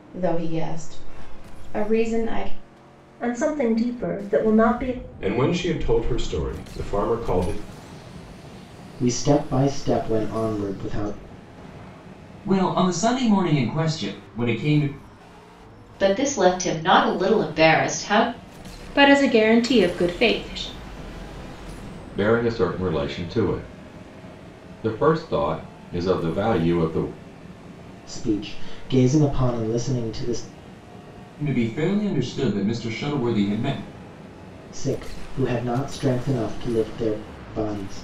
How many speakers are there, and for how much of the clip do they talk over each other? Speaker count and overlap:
eight, no overlap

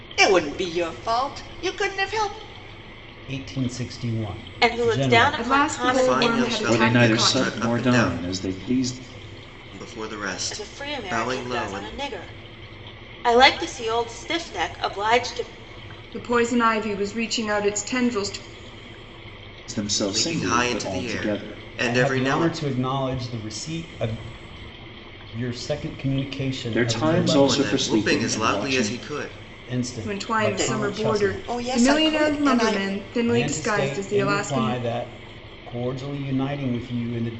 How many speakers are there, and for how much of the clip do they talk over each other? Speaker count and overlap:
six, about 37%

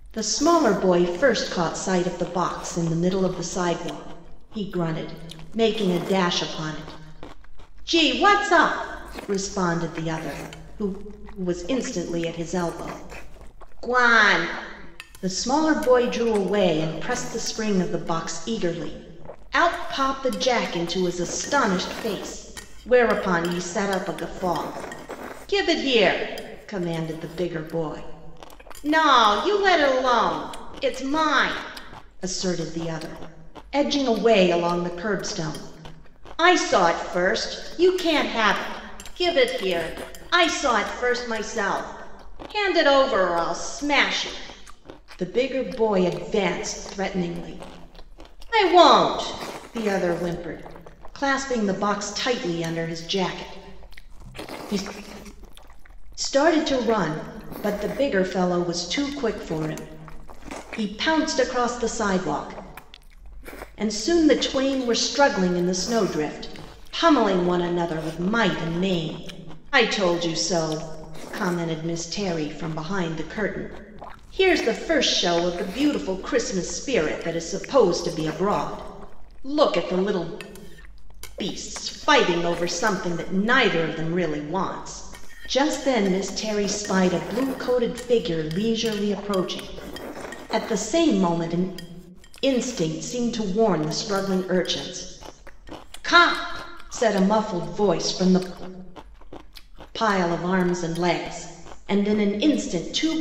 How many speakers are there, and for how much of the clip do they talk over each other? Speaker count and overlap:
one, no overlap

